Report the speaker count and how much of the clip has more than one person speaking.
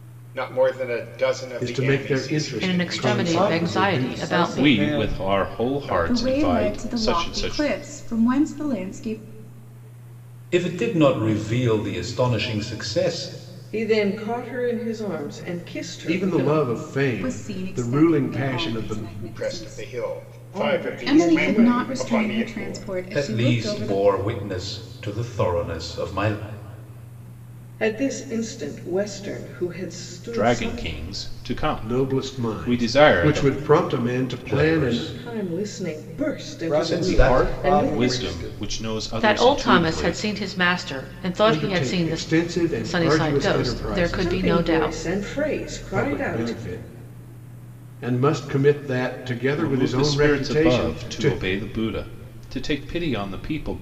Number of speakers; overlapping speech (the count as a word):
eight, about 48%